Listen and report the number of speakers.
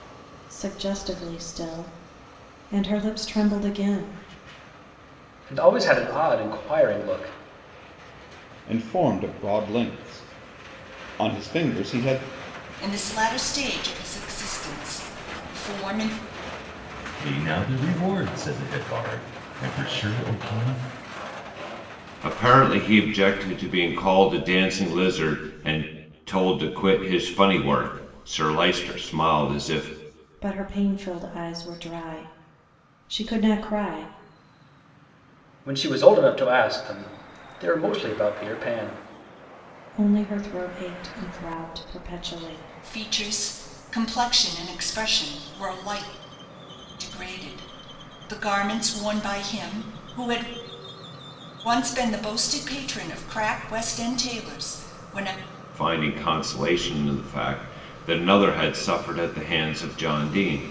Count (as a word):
six